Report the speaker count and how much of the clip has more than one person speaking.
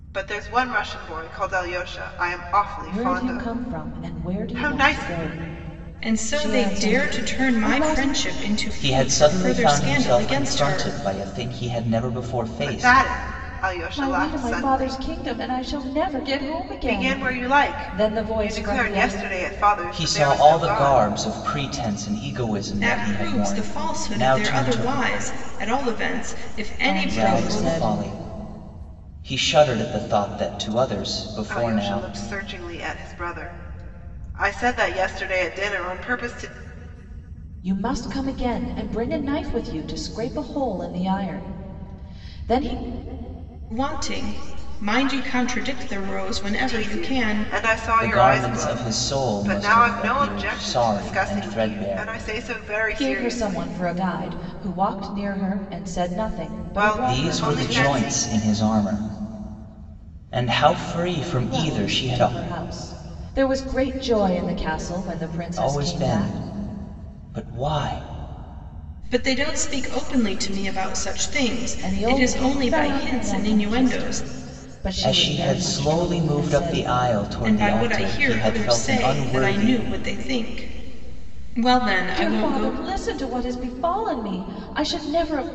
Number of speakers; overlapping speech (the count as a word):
four, about 37%